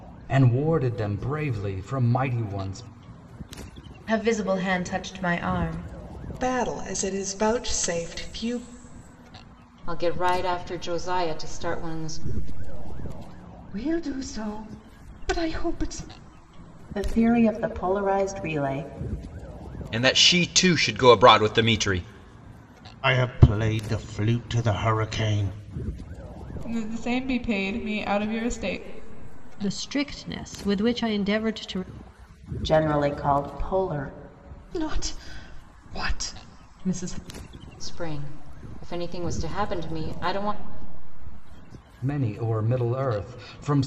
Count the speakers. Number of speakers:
10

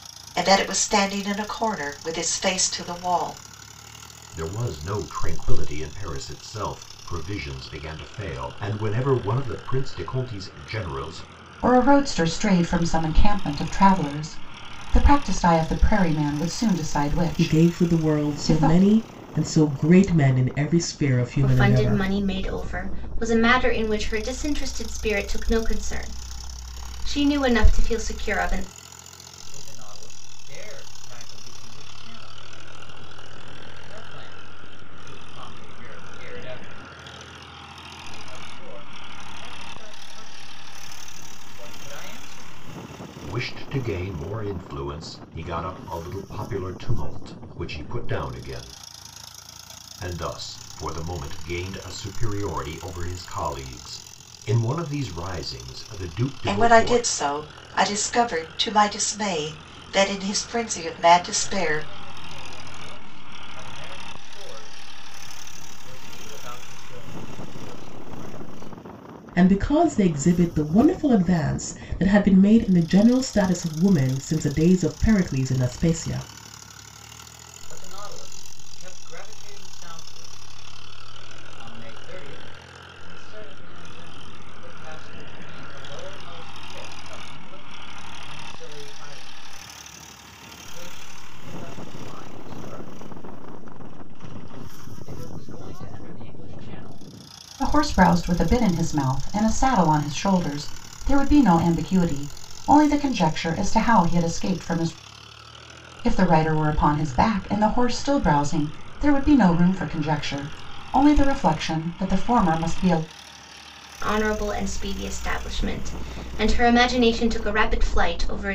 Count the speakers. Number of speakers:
6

